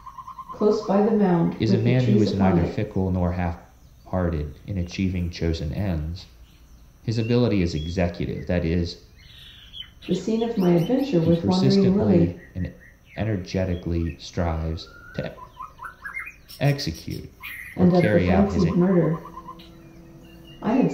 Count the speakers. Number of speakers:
two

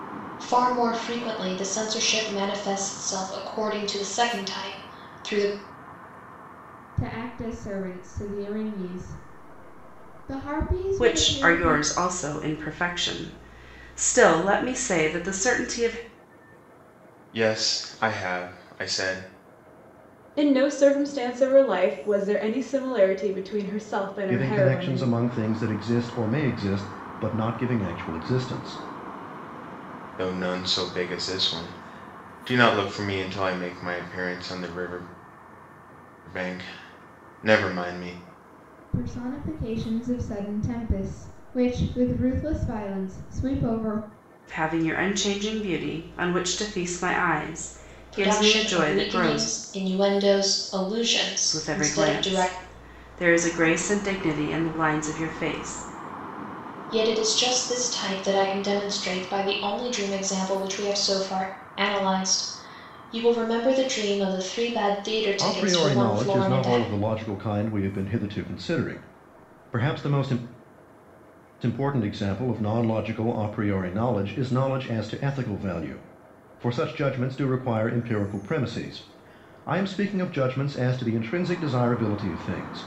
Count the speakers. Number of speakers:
six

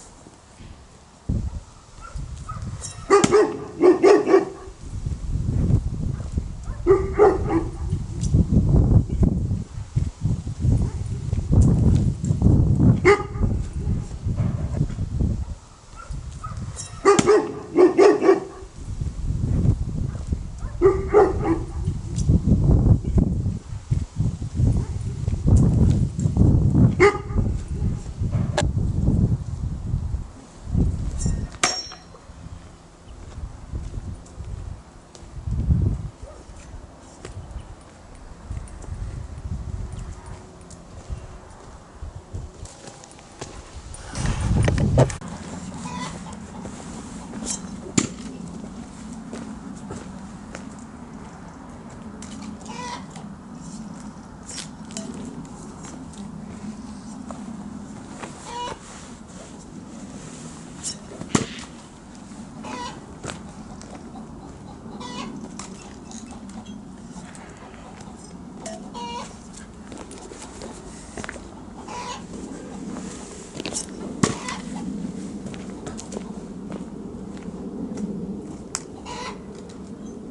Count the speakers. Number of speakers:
zero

